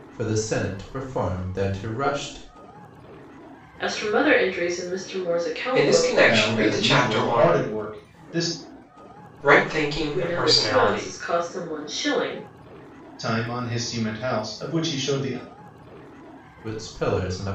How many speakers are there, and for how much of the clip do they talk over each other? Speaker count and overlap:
4, about 16%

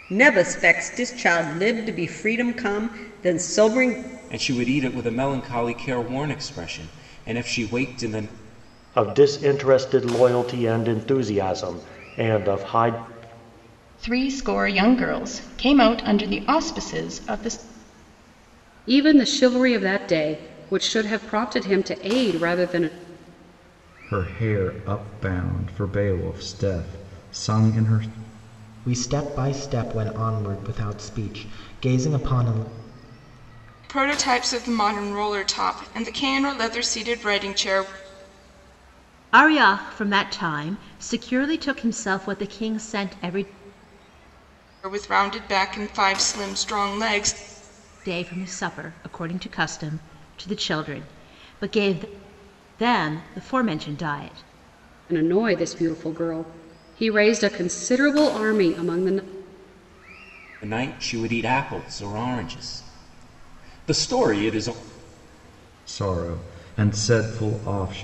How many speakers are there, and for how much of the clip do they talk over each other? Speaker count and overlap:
9, no overlap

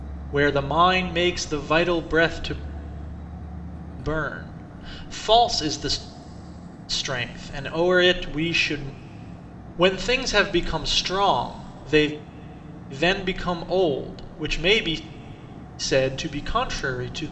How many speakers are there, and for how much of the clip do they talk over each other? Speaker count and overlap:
1, no overlap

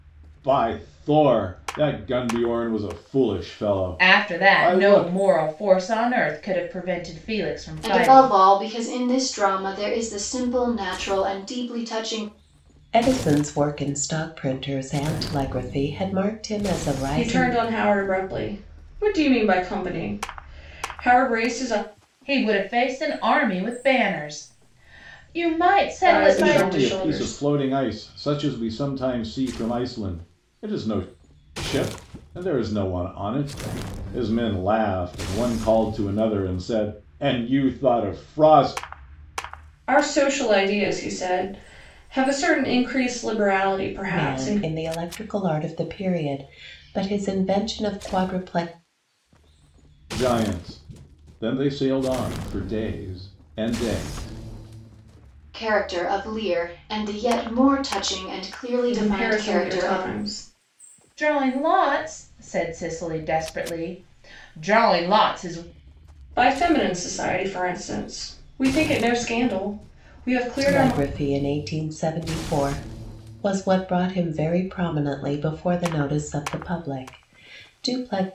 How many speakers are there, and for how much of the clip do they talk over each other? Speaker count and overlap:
5, about 7%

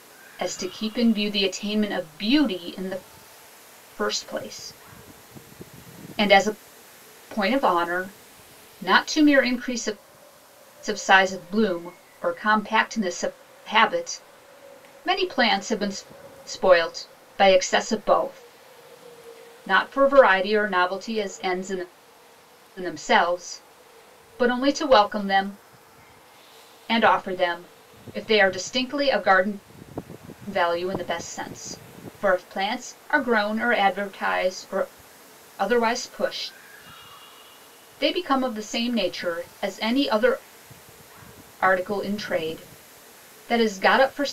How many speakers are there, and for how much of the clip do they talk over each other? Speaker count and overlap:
1, no overlap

